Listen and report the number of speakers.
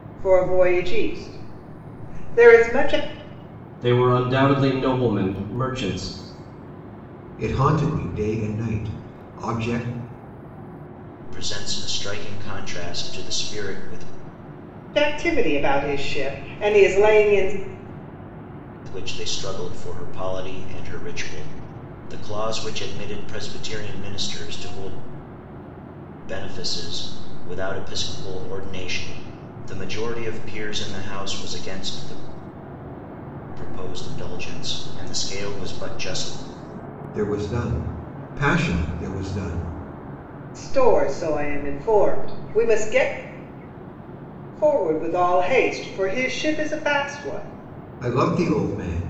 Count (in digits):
4